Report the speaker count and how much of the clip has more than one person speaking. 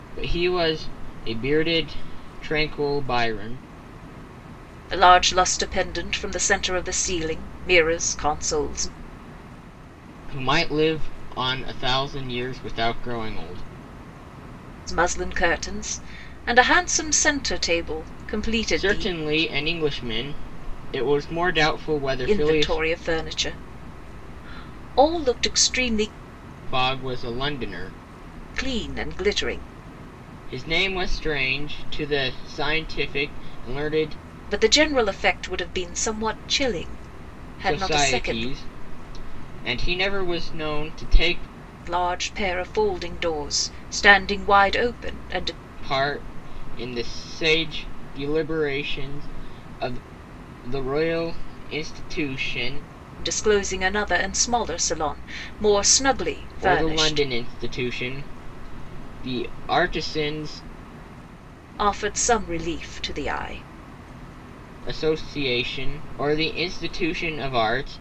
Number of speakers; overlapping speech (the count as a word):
two, about 4%